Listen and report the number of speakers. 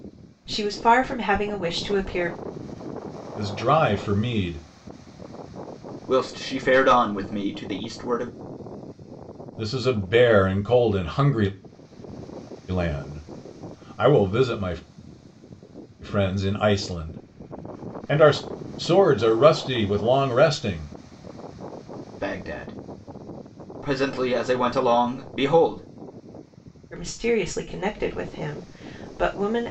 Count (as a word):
three